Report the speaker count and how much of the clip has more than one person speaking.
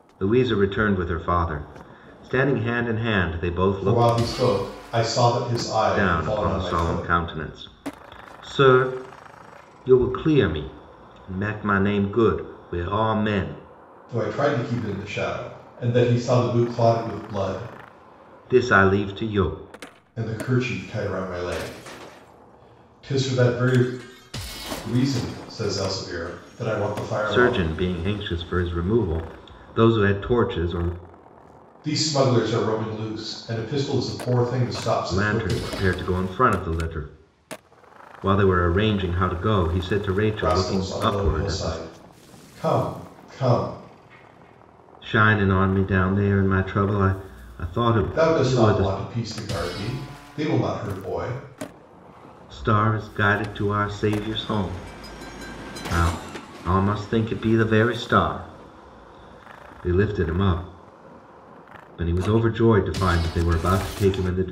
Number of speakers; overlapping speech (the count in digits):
2, about 8%